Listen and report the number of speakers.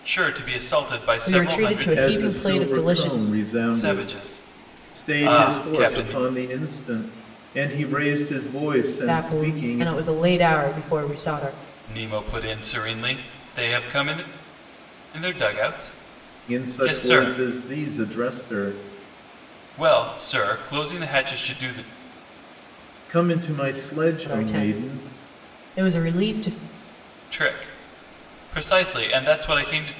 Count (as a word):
three